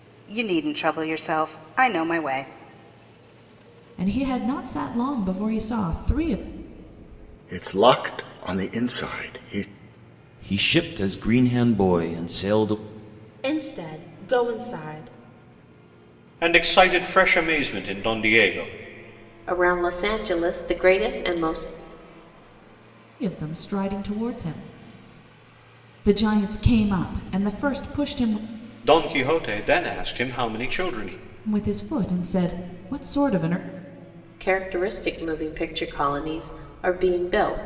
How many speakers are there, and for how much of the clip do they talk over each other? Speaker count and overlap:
seven, no overlap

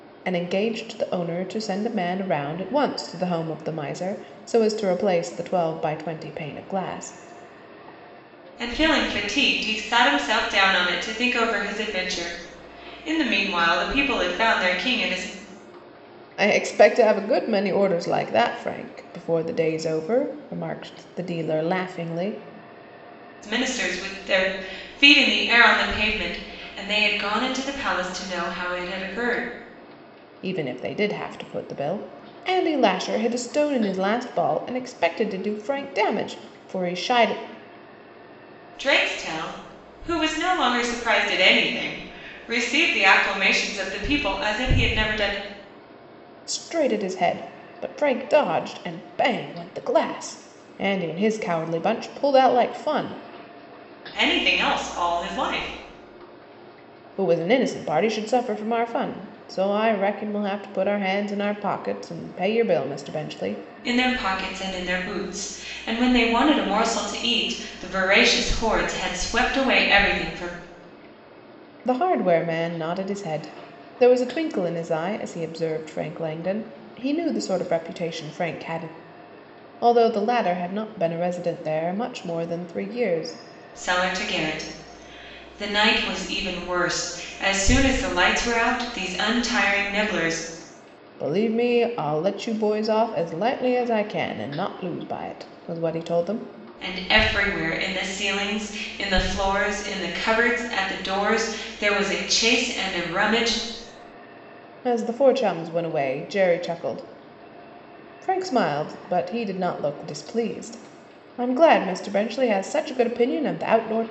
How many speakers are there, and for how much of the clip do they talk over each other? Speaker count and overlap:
two, no overlap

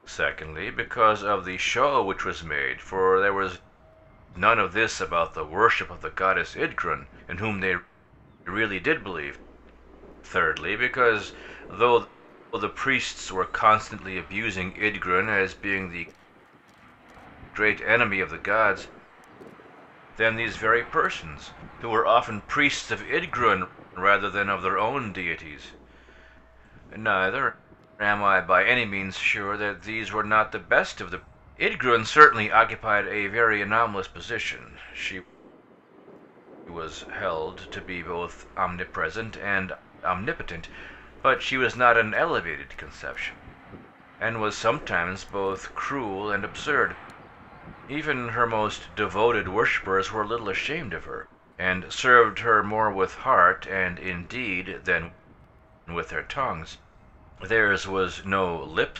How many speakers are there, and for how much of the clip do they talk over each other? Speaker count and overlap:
one, no overlap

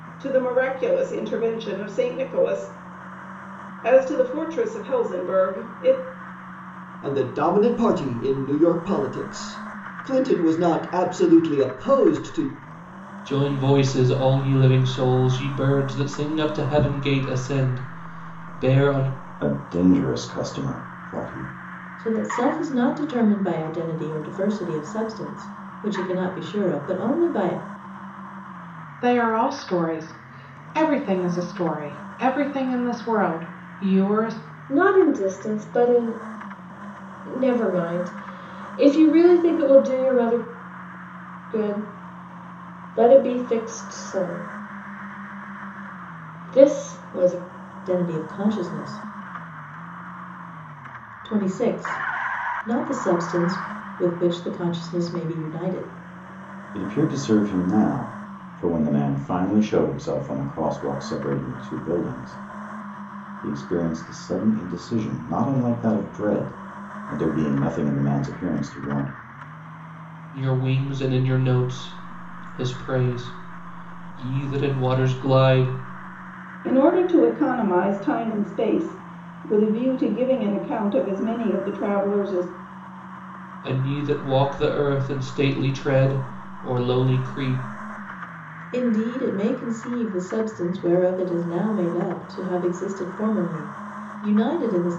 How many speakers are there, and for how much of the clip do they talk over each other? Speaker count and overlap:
seven, no overlap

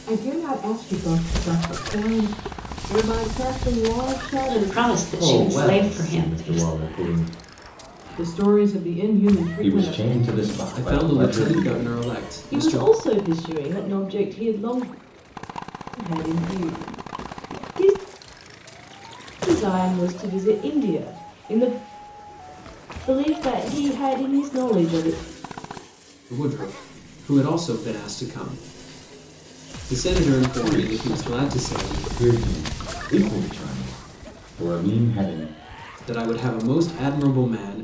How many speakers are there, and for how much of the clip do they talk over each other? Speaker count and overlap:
eight, about 15%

